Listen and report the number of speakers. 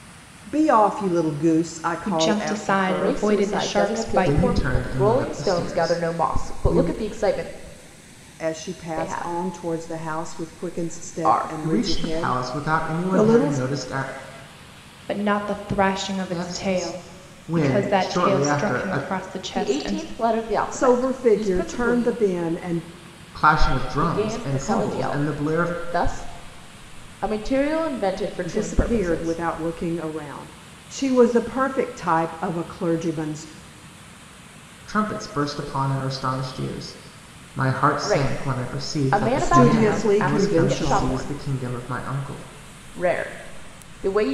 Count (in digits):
4